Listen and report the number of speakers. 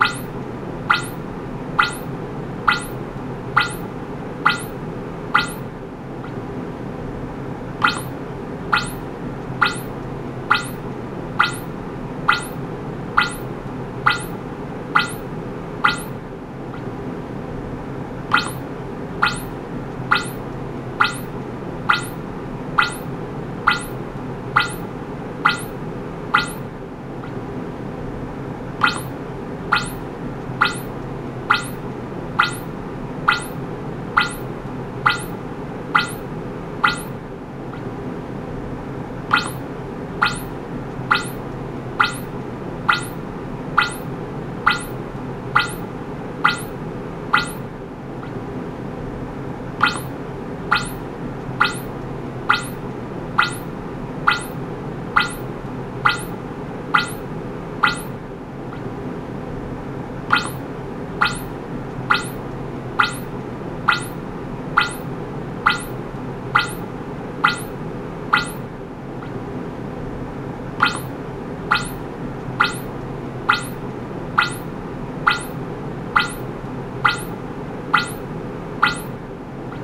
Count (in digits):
0